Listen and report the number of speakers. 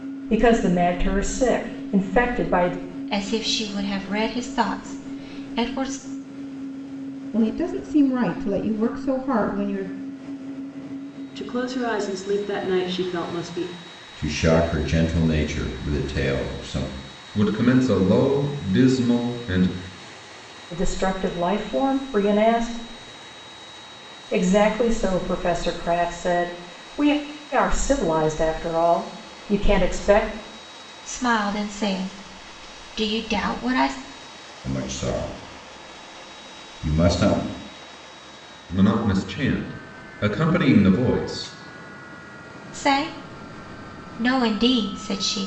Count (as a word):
six